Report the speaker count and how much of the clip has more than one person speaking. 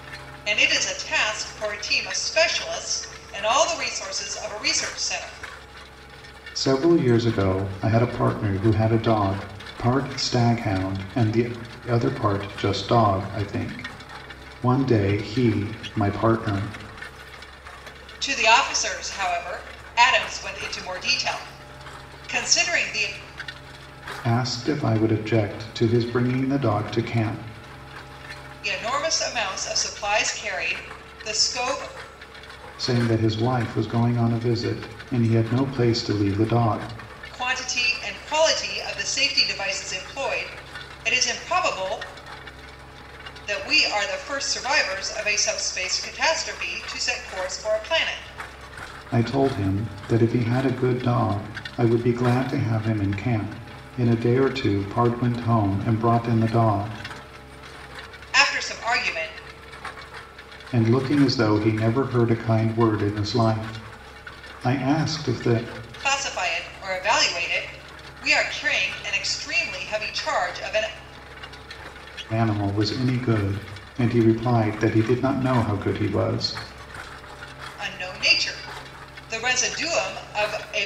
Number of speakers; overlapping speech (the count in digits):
2, no overlap